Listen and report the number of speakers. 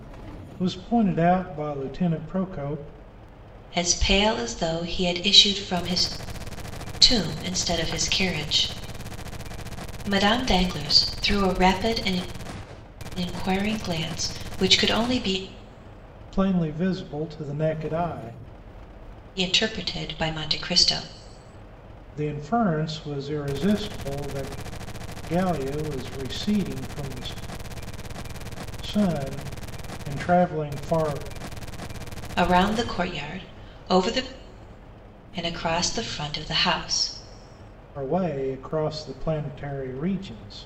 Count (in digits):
2